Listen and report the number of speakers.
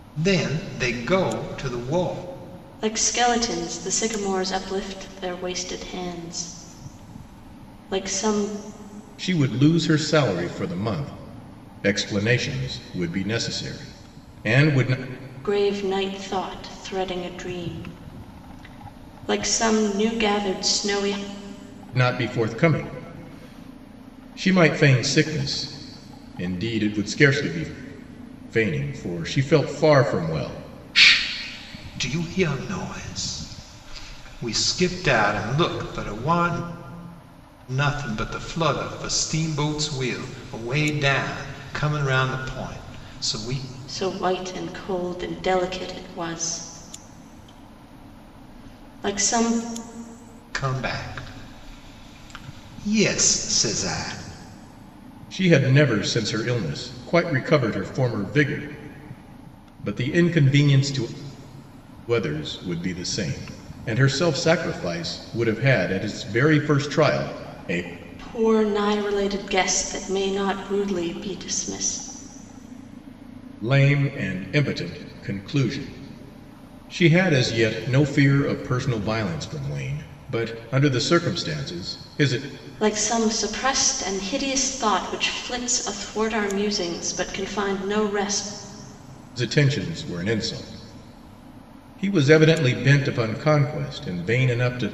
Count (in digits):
3